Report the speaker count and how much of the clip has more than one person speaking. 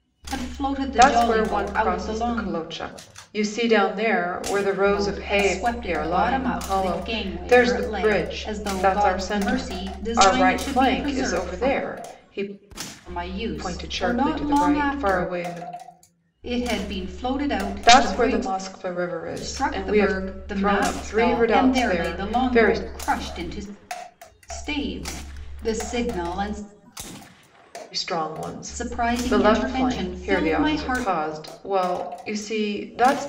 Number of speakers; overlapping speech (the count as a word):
two, about 48%